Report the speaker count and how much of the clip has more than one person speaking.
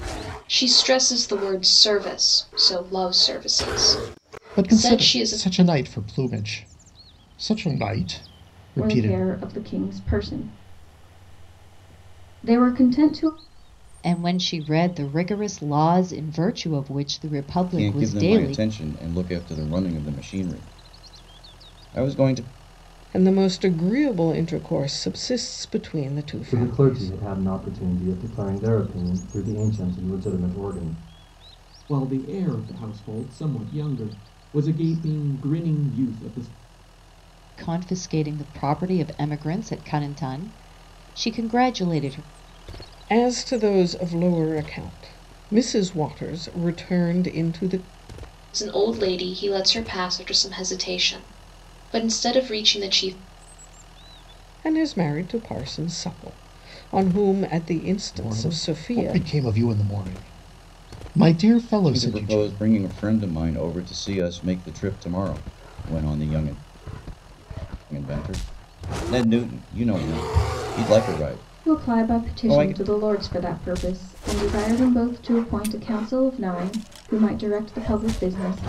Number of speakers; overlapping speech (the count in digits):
8, about 8%